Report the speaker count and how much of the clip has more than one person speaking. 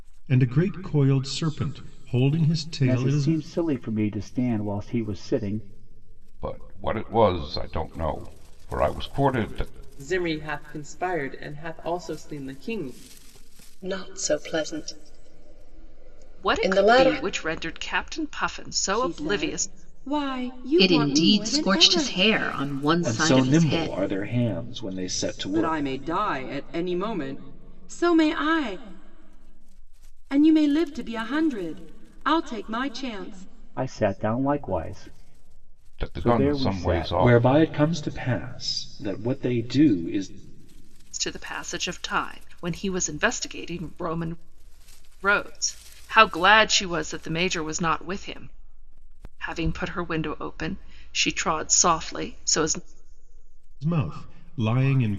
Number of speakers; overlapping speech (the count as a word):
nine, about 12%